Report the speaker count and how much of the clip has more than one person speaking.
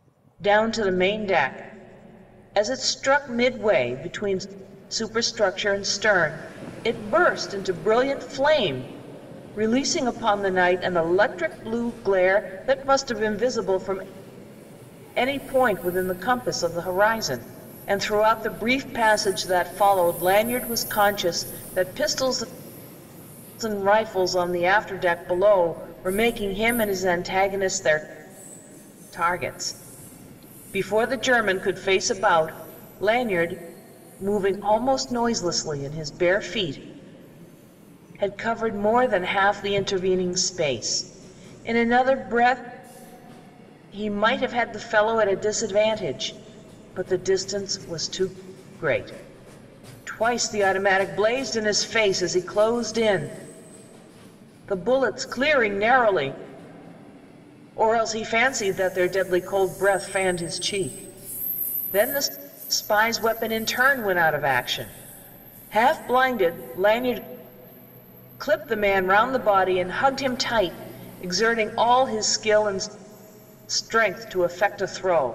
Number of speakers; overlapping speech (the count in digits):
1, no overlap